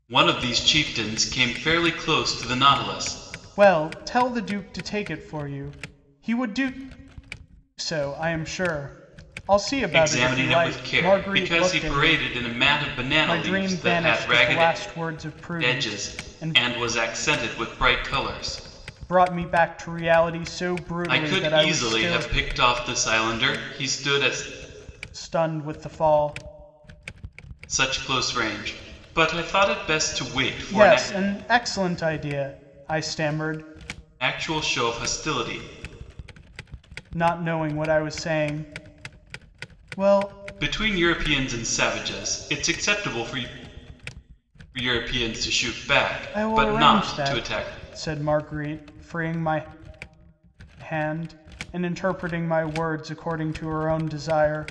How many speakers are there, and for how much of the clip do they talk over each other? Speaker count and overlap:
two, about 14%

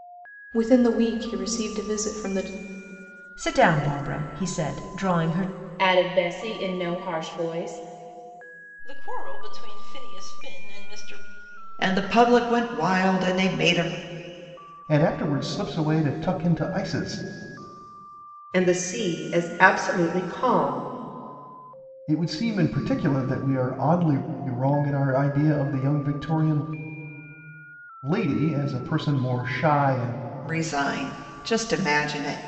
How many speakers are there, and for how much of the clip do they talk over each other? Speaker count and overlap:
seven, no overlap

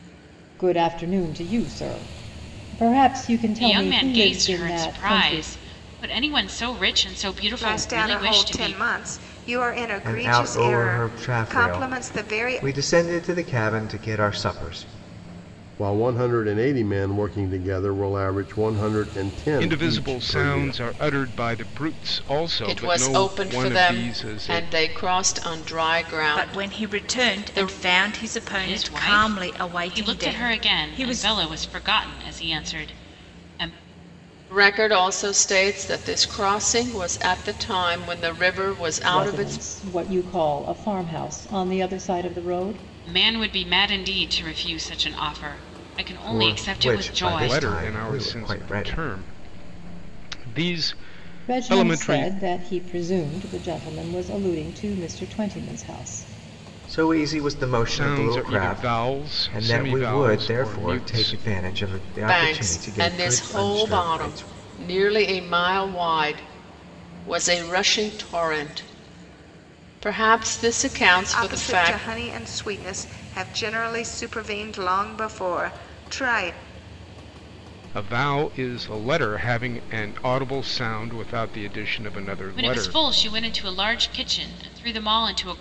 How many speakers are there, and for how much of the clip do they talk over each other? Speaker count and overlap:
eight, about 28%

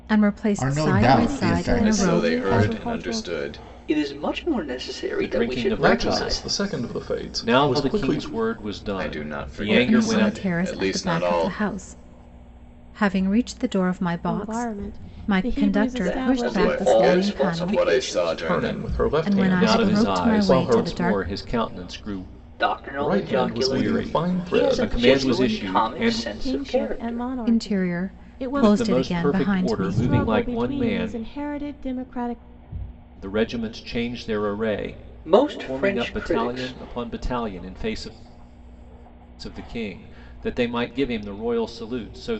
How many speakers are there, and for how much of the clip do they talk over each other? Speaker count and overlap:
seven, about 57%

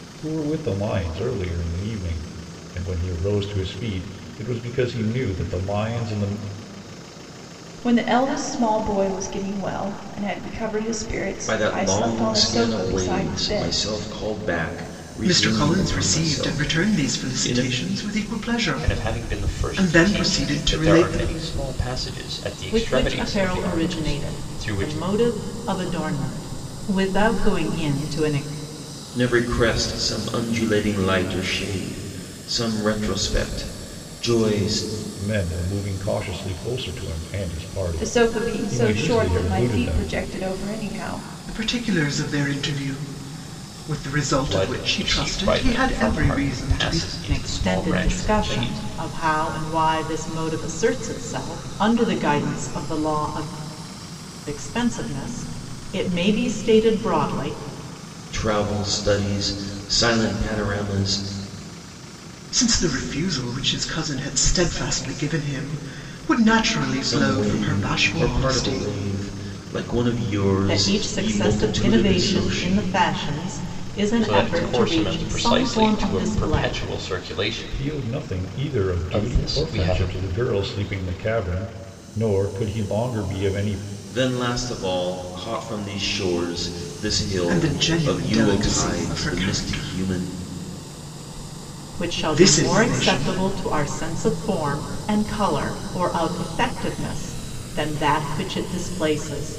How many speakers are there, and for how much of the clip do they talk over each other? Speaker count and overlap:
six, about 30%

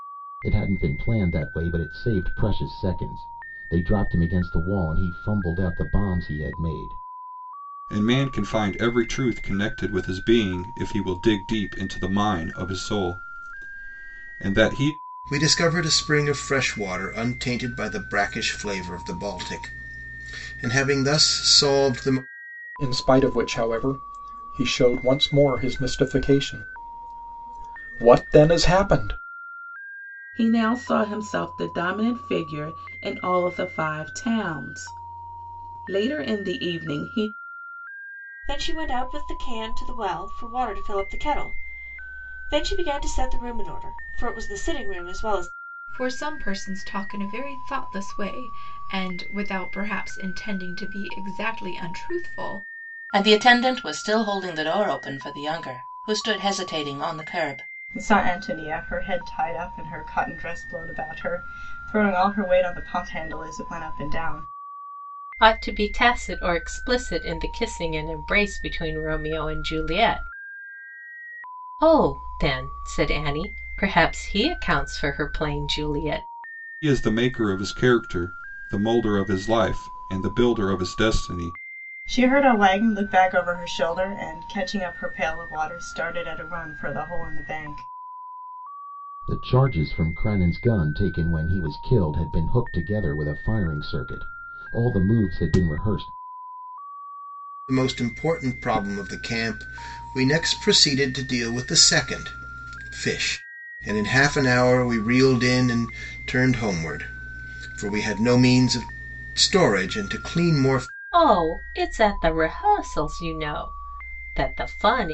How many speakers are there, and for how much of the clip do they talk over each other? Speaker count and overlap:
ten, no overlap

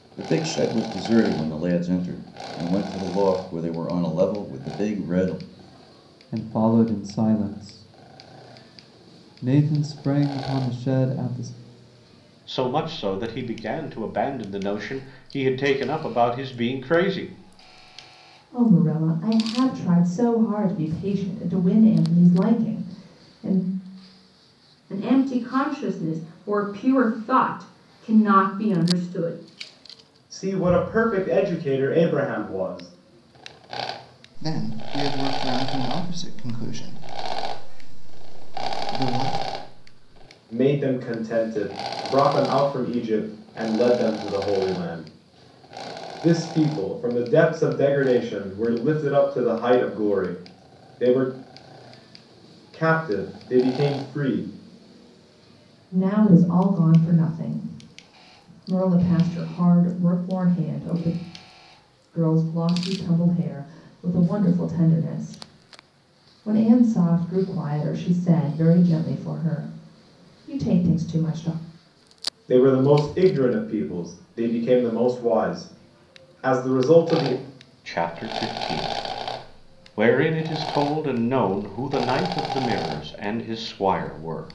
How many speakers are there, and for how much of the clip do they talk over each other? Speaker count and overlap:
seven, no overlap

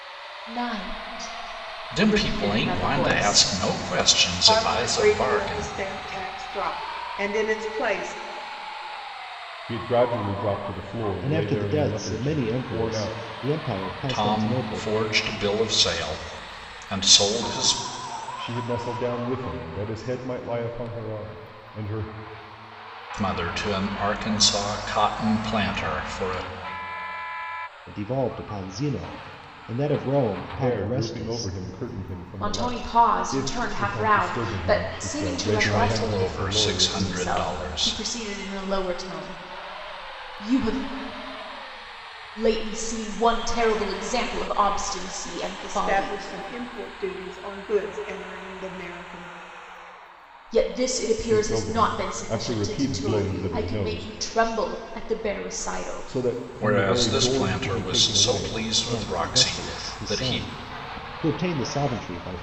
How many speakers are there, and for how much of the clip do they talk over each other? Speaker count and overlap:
five, about 32%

